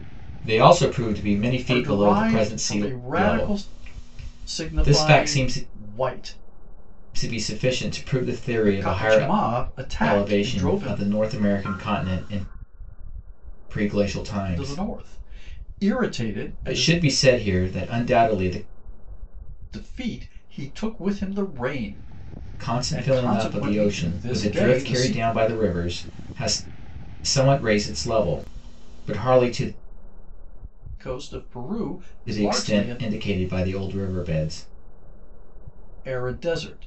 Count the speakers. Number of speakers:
two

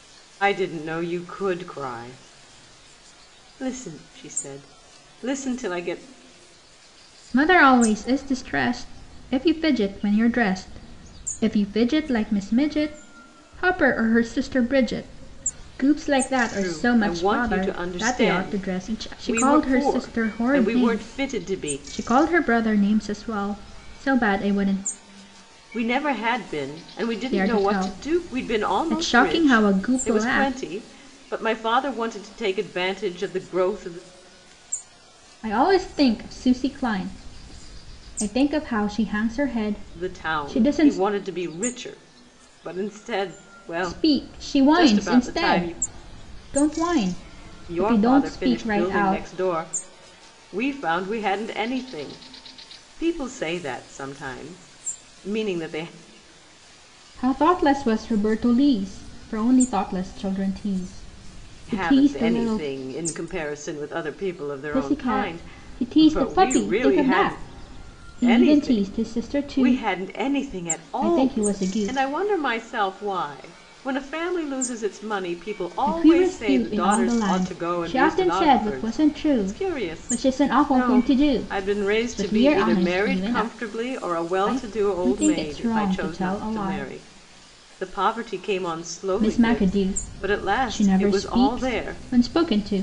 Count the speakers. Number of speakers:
two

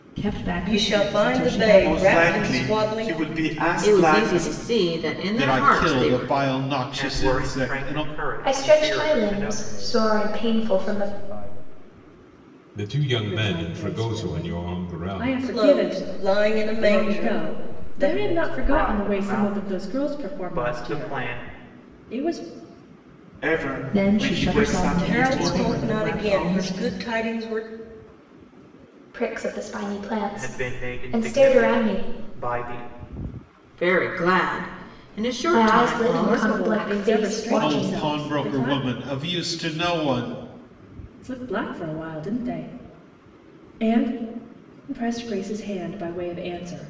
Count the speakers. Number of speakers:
ten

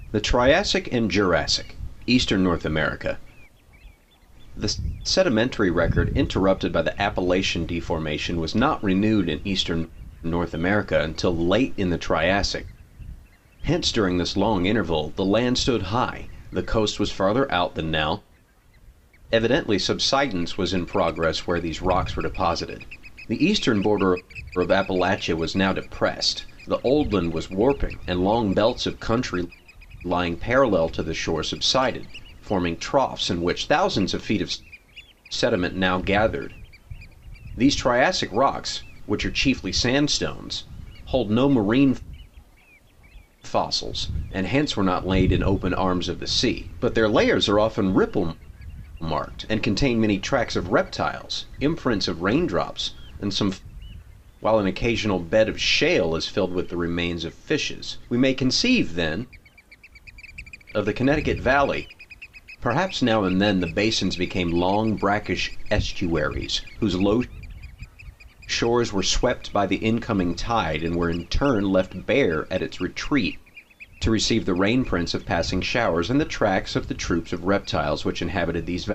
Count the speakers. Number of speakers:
one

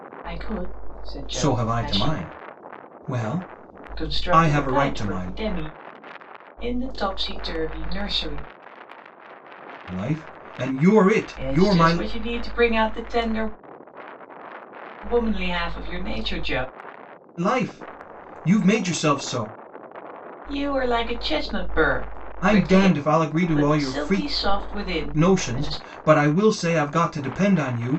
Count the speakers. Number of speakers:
two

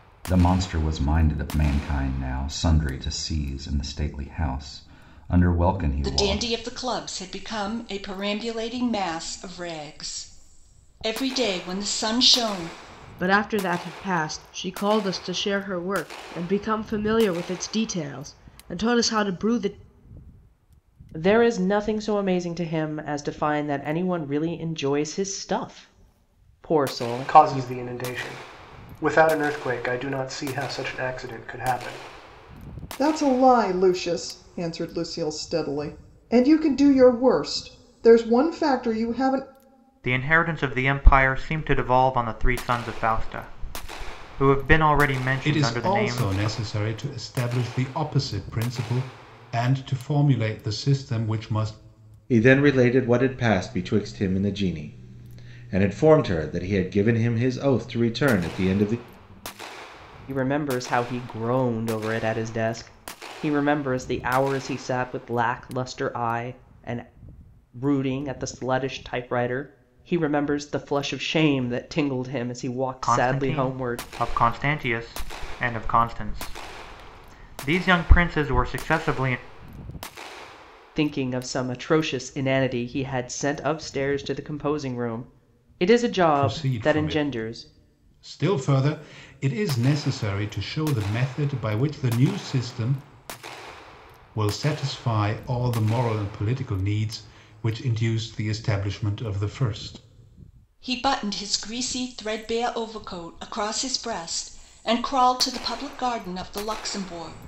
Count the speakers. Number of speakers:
nine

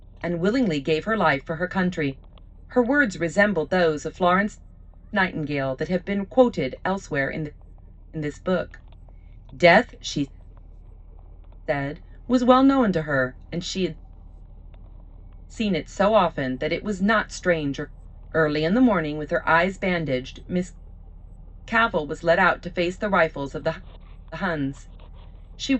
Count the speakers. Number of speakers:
one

